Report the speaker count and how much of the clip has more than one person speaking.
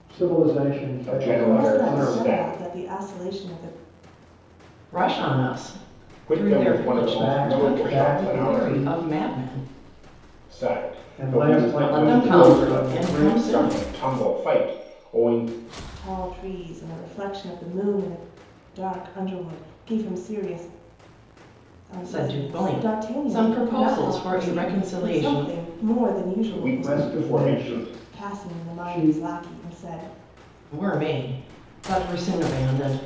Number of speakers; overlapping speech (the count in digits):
4, about 39%